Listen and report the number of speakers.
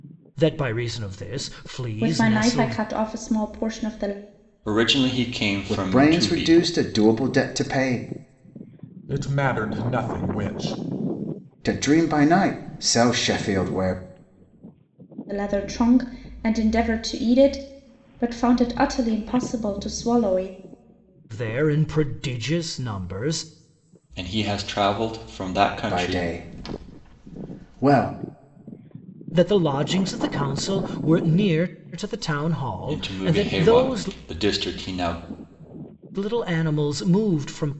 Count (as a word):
five